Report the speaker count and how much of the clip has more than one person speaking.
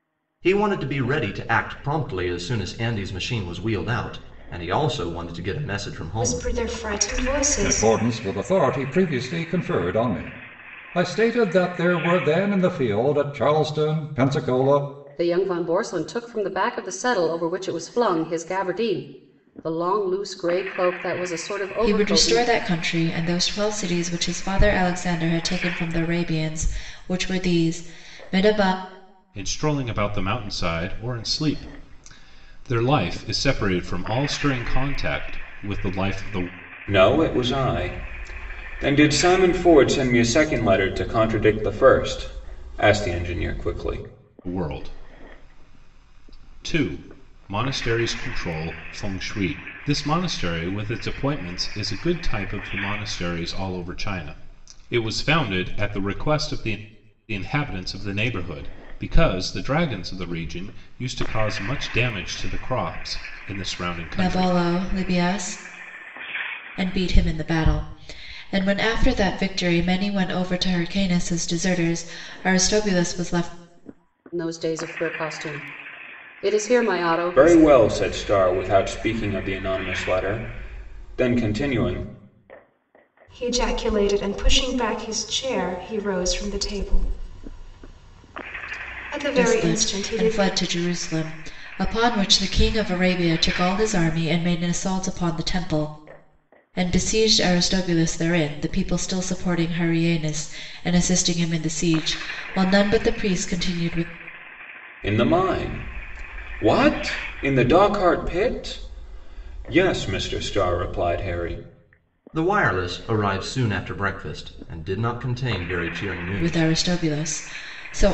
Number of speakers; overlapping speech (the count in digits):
7, about 3%